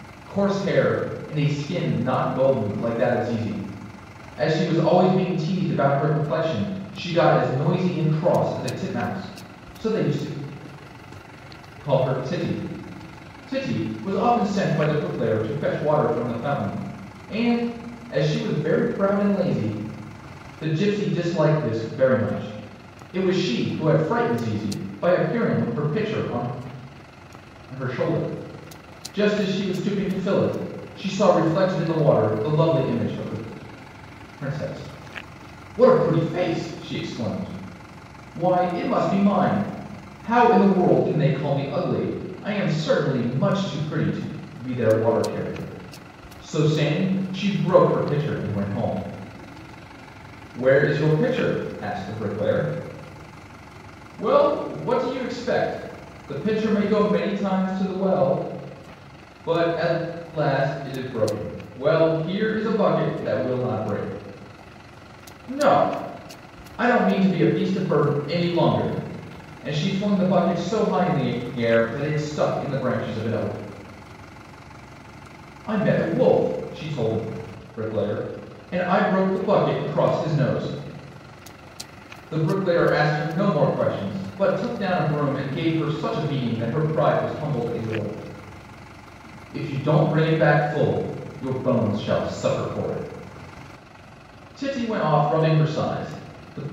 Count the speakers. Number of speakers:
one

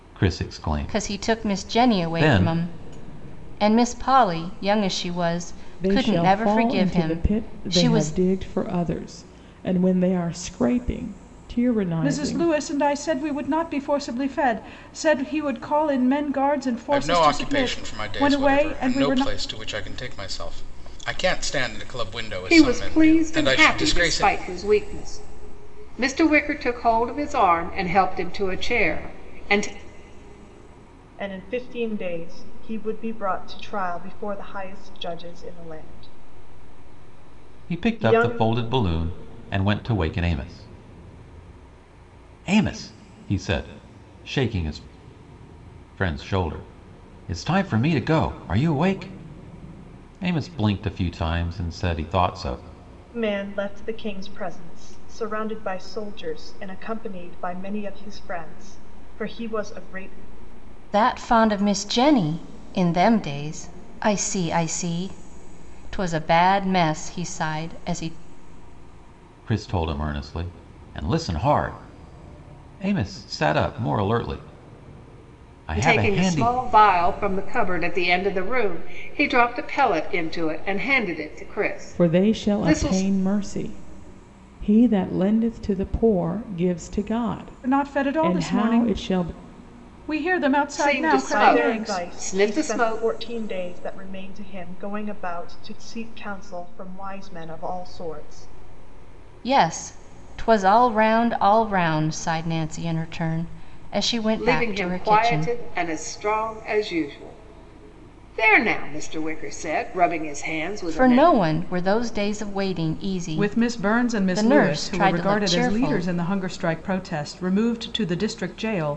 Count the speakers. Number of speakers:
seven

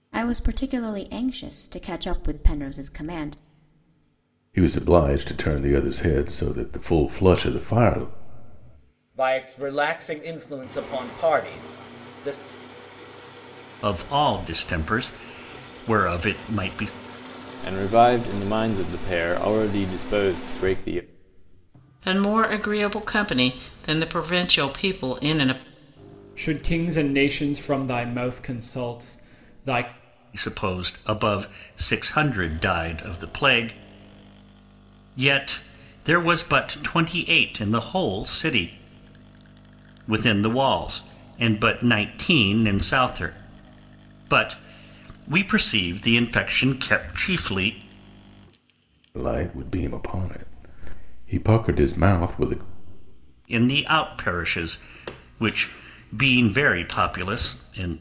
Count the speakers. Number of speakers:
seven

